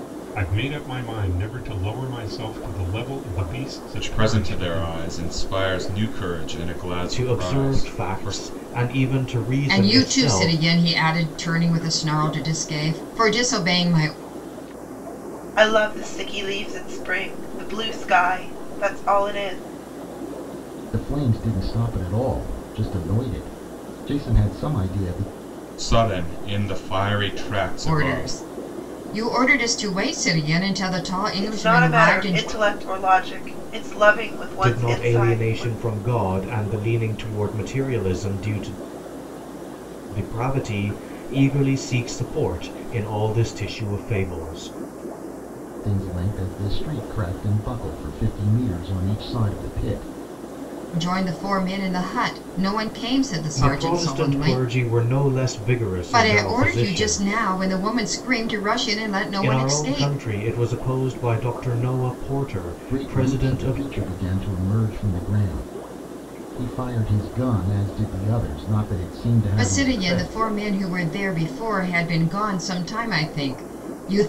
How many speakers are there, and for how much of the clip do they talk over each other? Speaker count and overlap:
6, about 15%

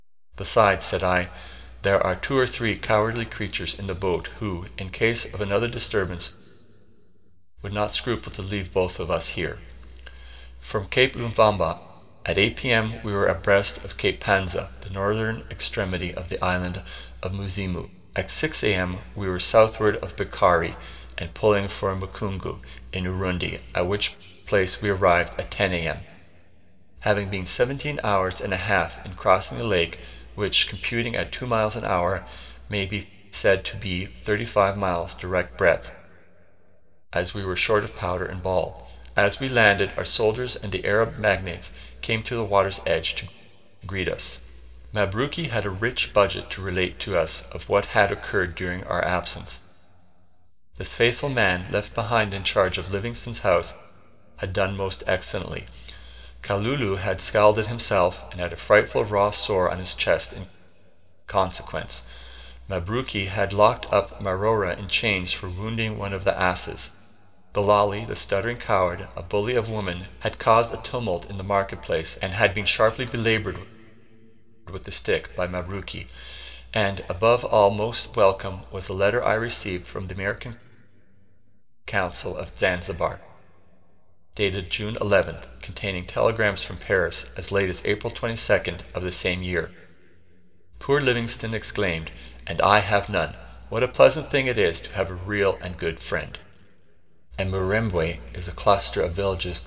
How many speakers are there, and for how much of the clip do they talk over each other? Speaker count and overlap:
1, no overlap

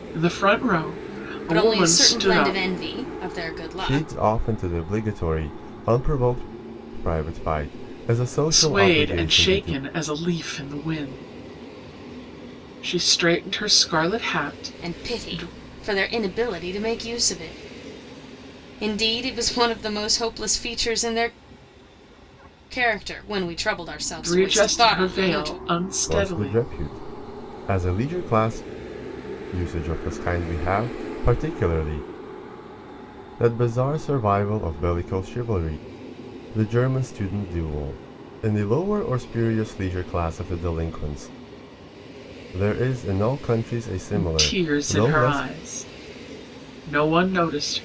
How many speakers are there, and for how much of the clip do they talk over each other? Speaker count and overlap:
3, about 15%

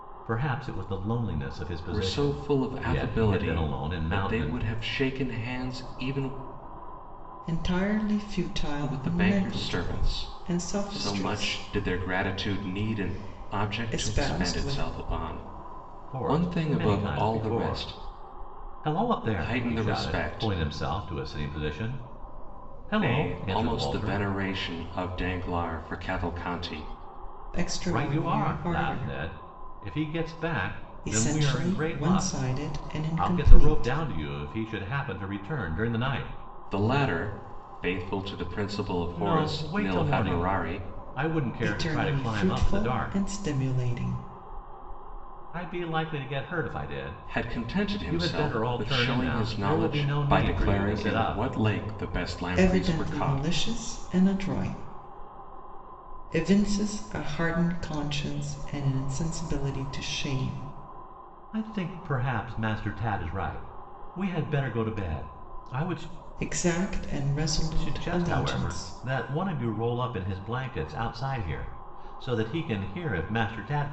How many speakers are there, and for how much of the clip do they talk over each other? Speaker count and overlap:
3, about 35%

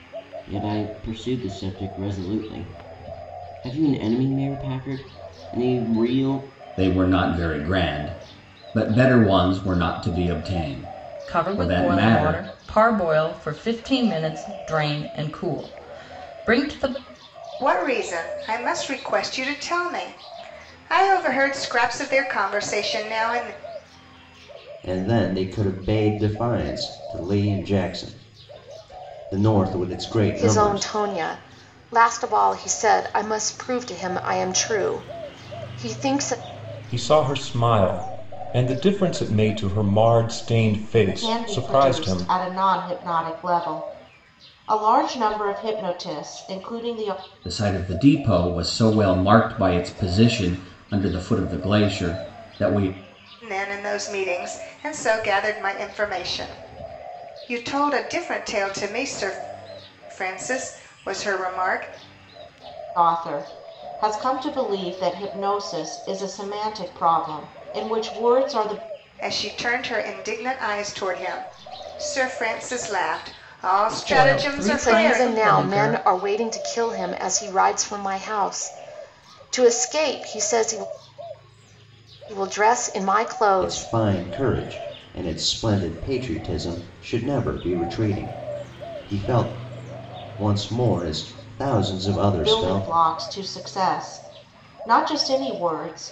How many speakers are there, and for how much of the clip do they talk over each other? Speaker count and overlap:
8, about 6%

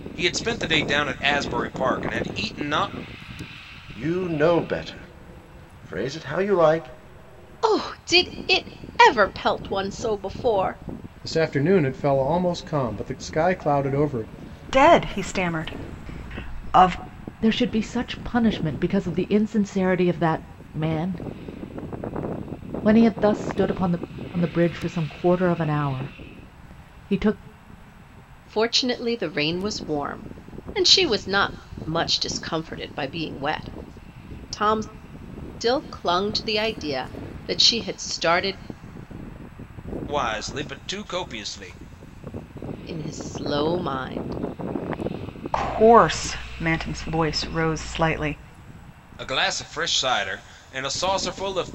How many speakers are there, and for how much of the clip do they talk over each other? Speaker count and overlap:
6, no overlap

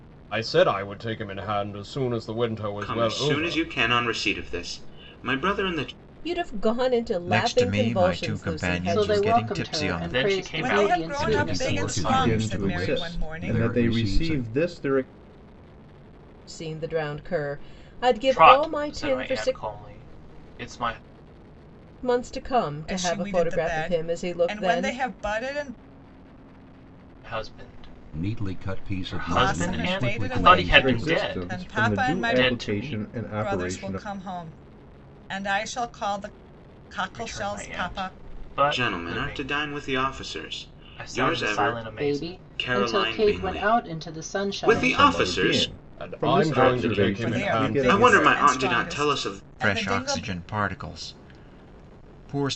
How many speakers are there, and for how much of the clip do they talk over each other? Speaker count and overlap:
9, about 53%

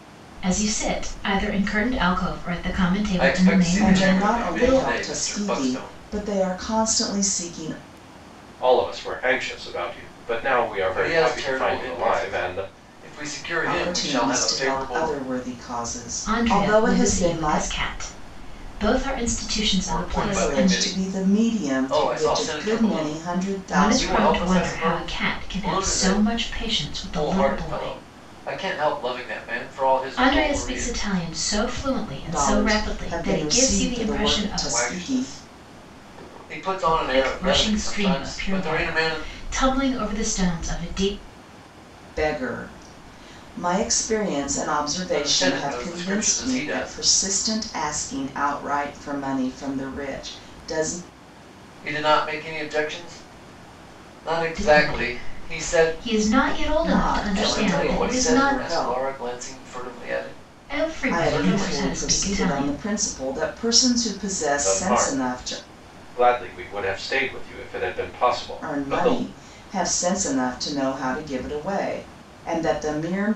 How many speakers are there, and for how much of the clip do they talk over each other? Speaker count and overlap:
4, about 40%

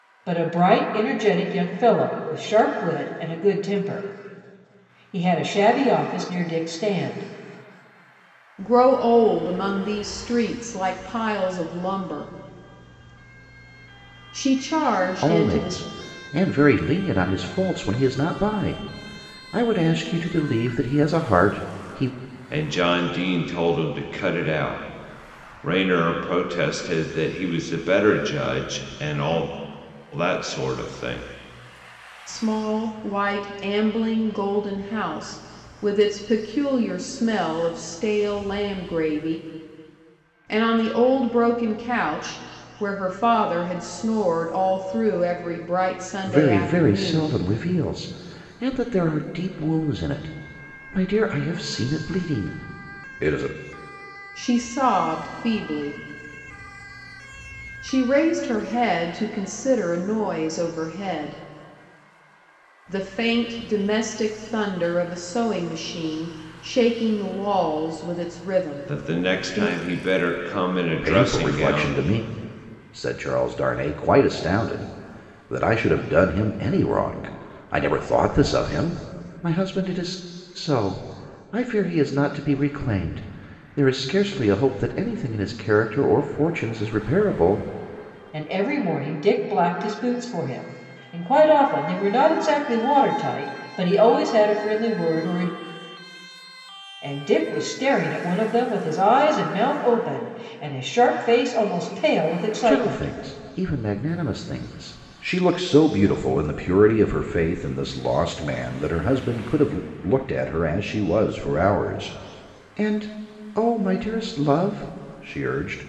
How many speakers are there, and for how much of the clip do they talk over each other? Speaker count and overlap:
4, about 4%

